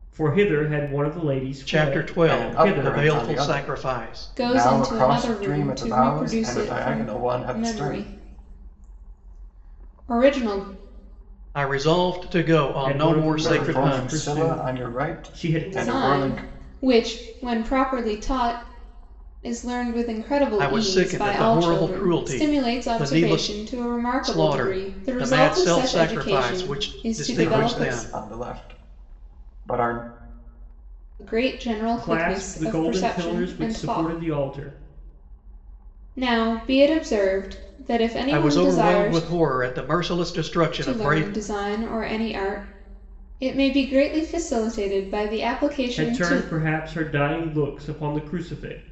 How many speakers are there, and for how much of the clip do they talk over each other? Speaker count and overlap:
4, about 42%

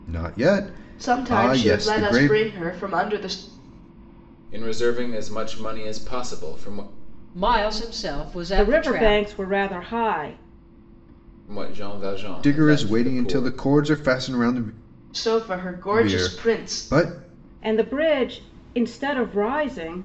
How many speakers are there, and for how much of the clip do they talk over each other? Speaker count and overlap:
5, about 22%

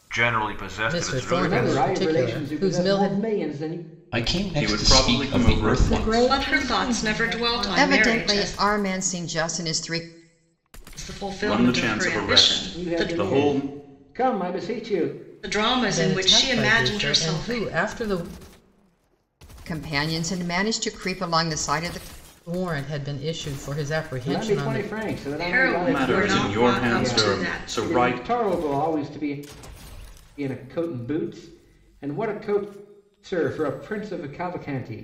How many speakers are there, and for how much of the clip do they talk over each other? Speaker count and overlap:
8, about 40%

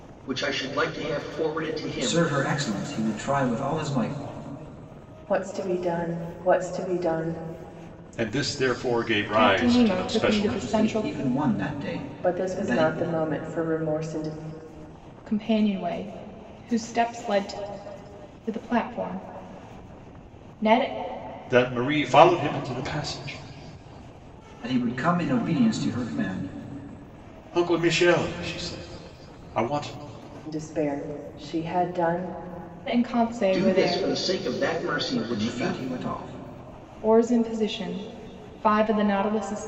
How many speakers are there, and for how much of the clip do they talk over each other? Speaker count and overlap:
5, about 11%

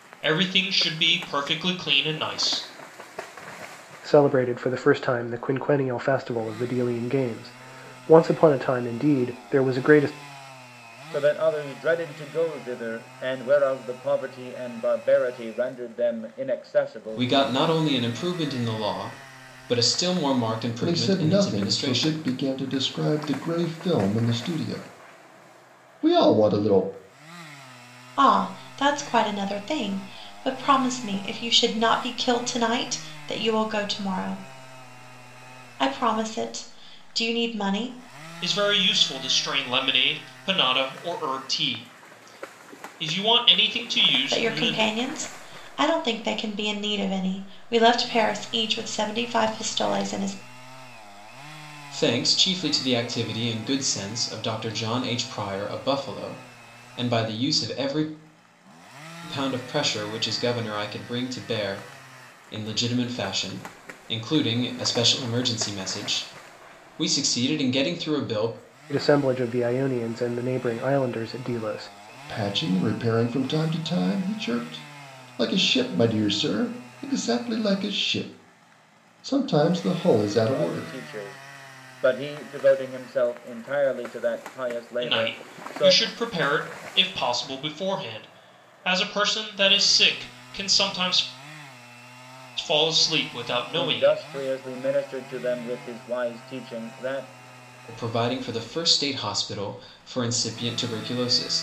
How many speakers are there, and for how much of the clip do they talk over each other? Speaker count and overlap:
6, about 4%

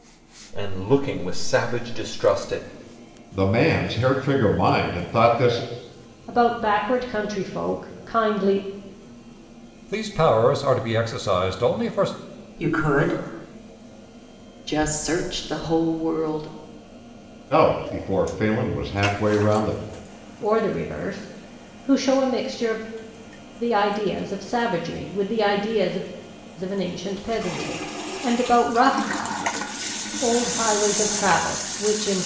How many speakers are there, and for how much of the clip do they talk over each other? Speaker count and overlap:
6, no overlap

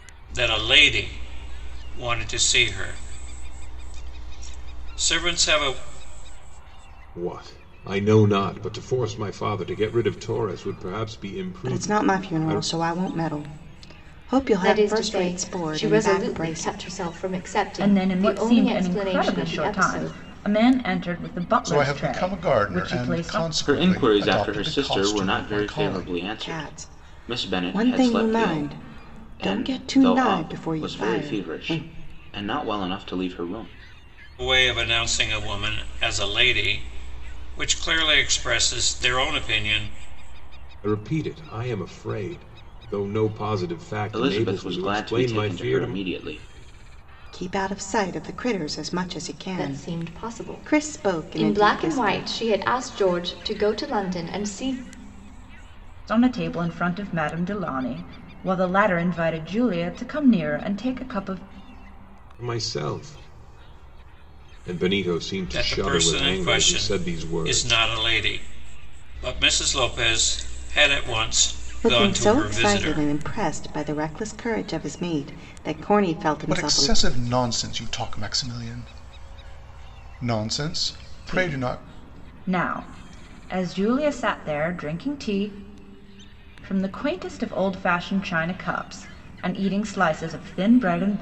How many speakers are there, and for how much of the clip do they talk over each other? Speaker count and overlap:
7, about 27%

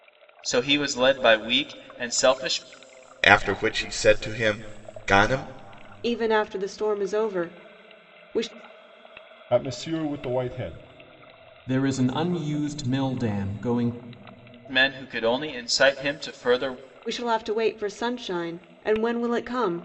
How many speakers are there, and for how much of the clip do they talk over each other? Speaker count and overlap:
5, no overlap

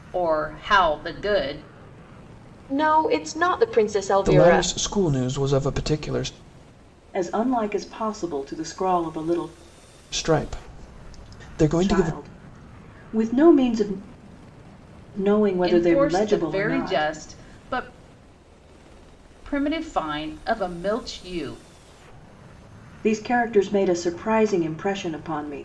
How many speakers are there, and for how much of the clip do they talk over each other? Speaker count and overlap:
4, about 9%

